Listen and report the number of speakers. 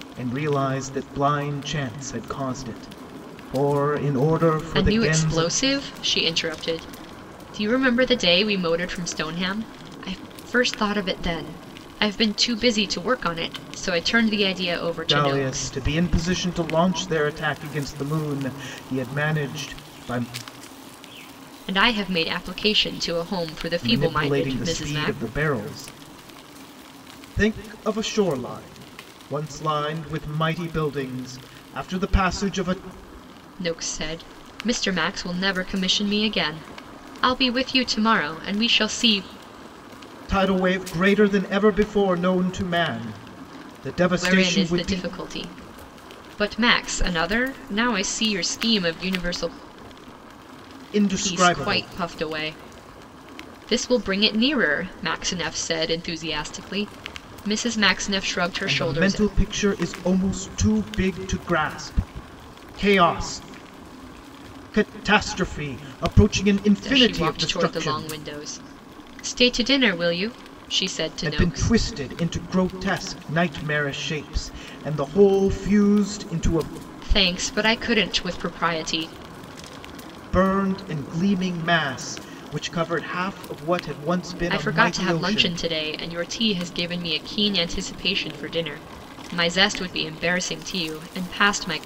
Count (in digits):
2